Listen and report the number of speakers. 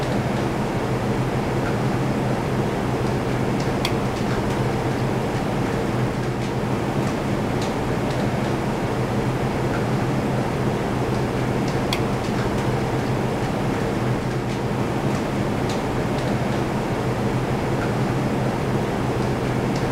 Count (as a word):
zero